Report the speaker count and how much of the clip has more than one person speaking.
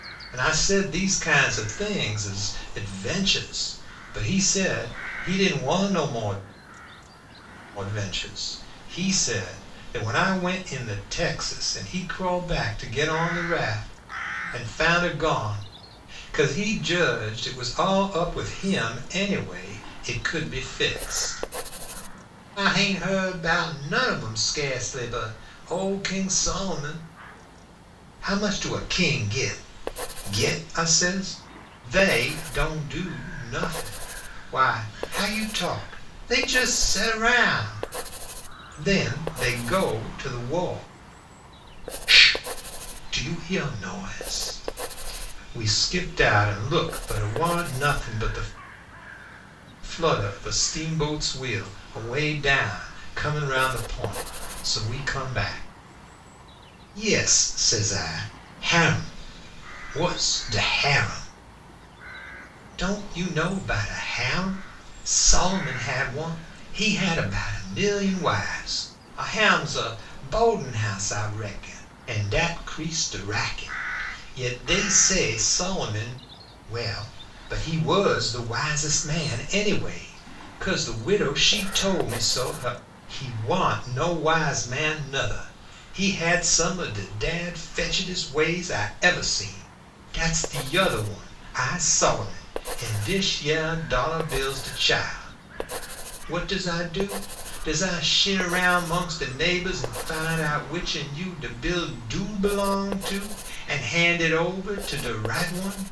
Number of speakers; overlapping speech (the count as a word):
one, no overlap